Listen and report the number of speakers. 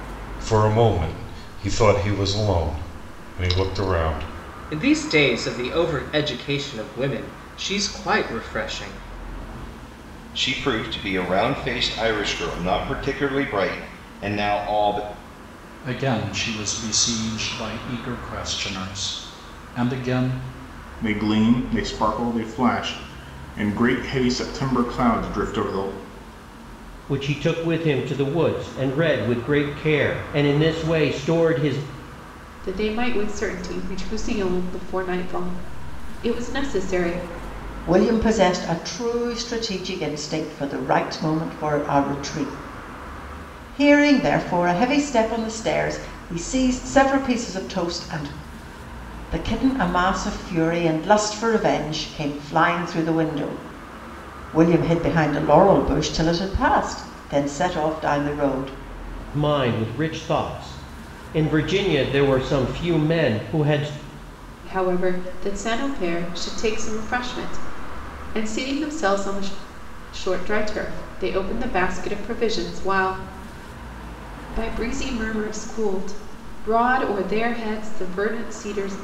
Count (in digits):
8